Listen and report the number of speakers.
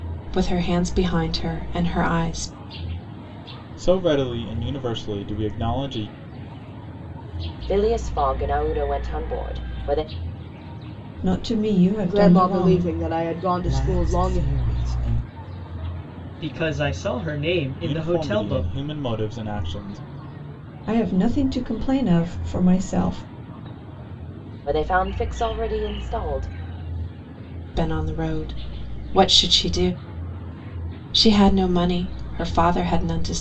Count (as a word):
seven